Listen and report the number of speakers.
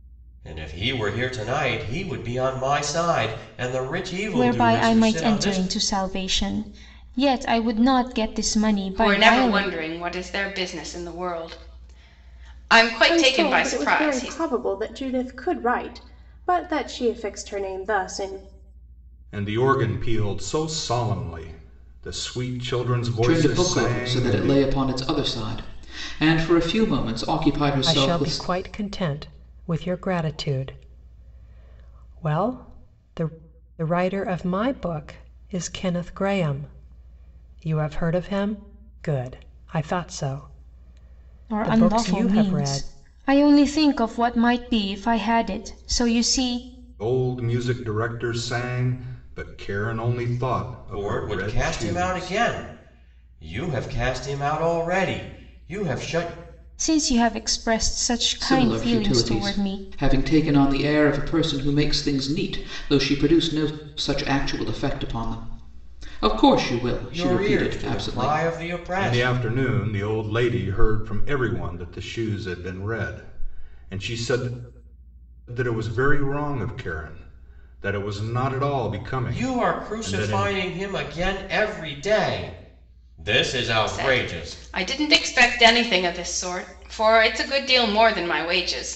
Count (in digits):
7